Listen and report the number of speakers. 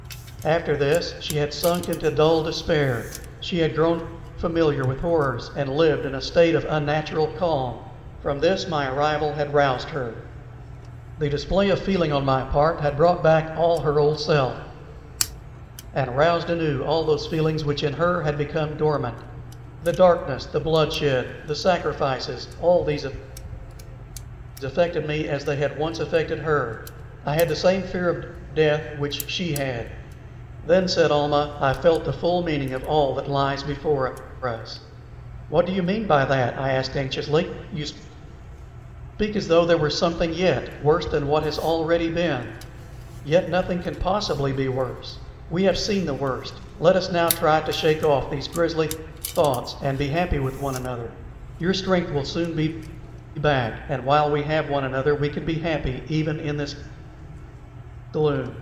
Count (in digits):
1